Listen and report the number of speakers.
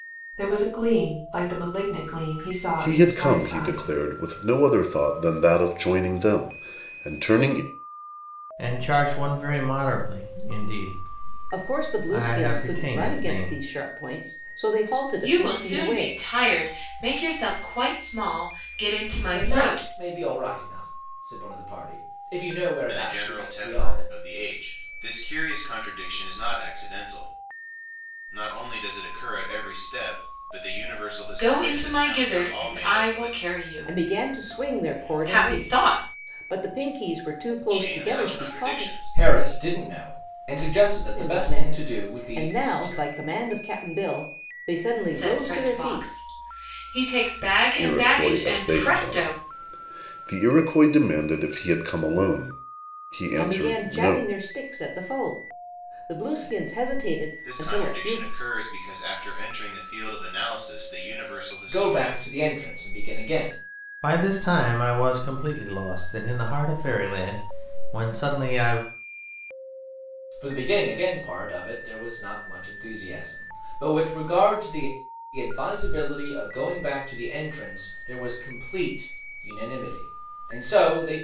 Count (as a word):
seven